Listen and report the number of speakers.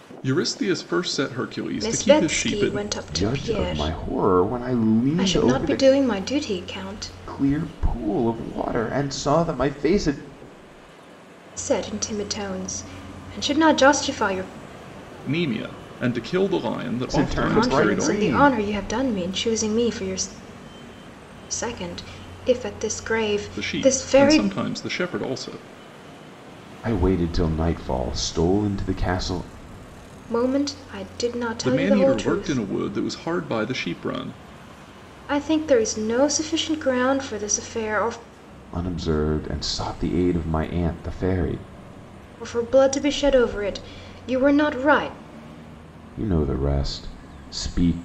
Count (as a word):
three